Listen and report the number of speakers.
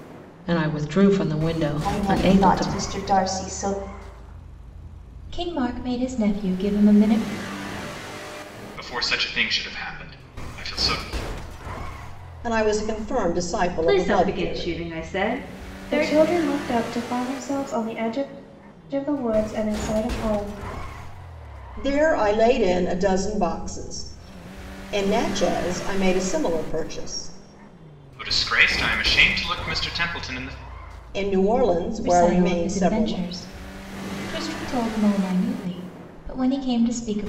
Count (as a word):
seven